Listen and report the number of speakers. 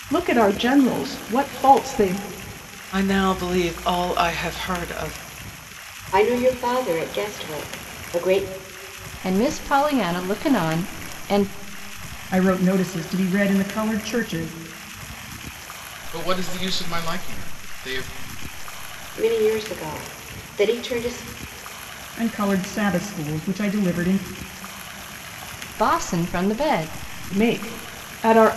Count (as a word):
six